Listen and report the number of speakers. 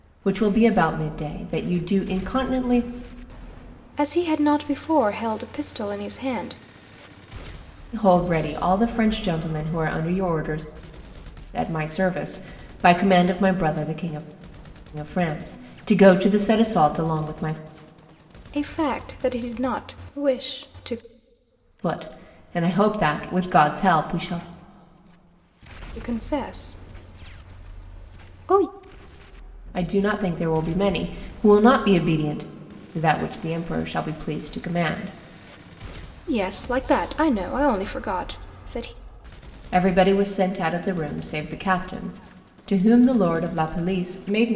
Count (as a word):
two